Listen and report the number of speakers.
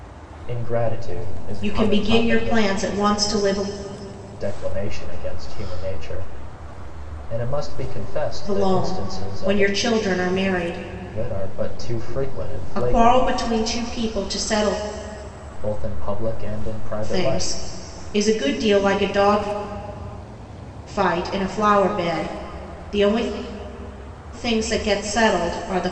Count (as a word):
two